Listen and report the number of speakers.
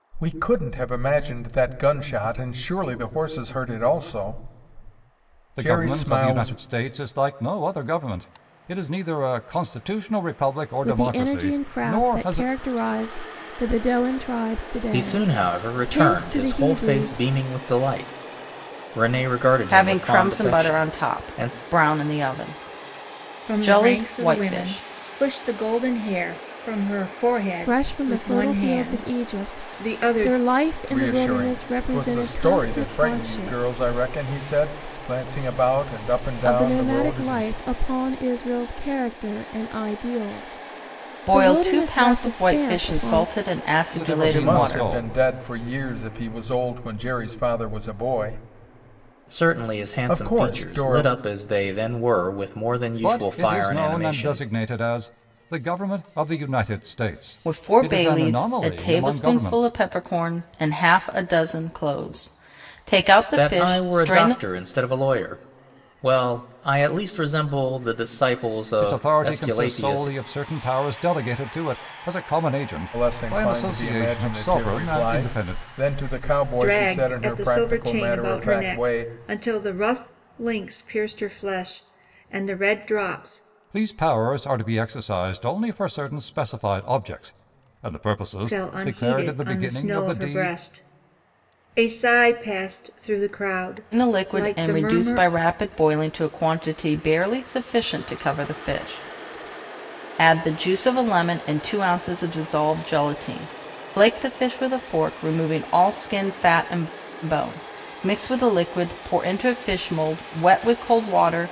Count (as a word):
six